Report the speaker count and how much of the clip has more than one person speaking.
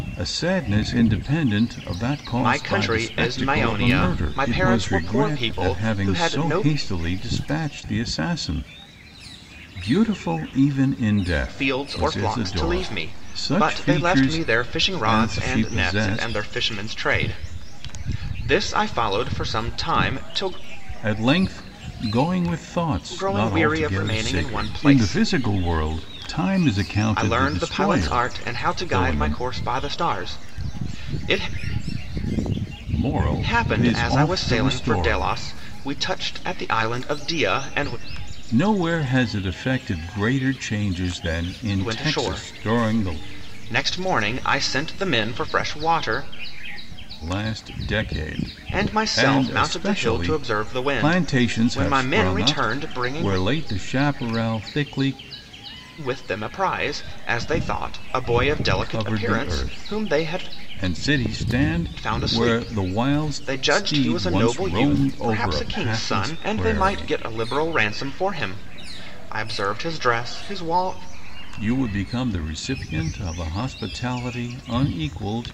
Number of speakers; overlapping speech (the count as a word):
two, about 36%